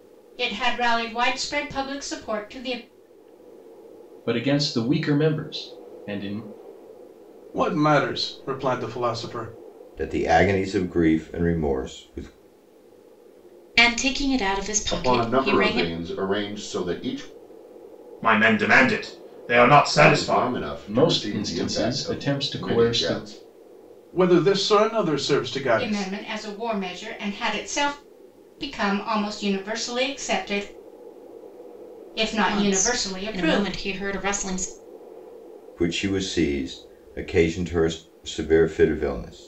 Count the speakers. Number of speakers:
7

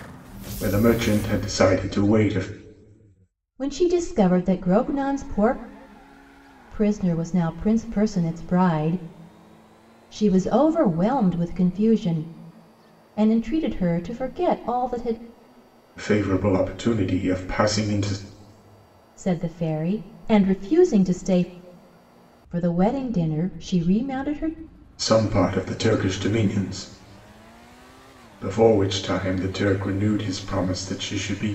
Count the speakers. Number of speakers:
2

